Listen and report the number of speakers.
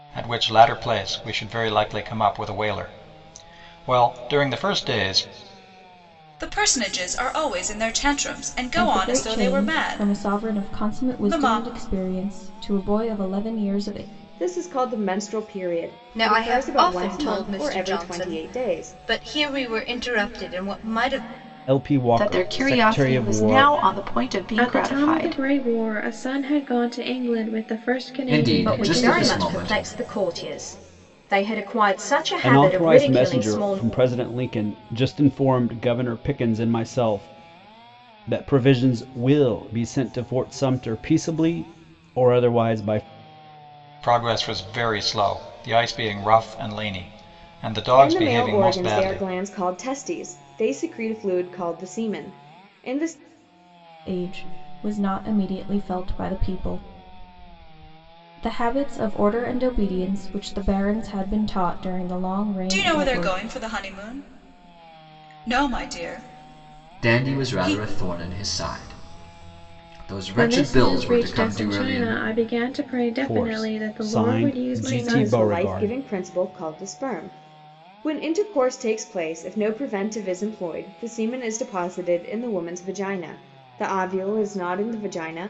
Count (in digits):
10